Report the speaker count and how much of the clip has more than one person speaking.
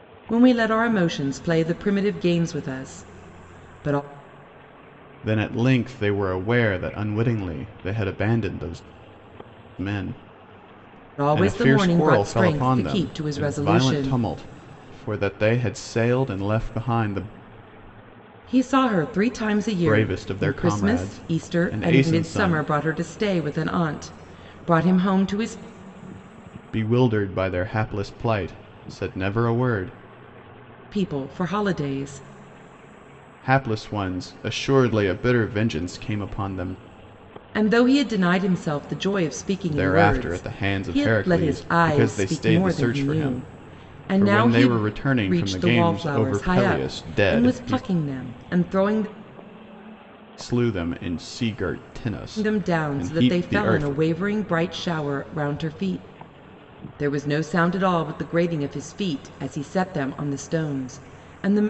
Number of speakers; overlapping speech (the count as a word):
two, about 24%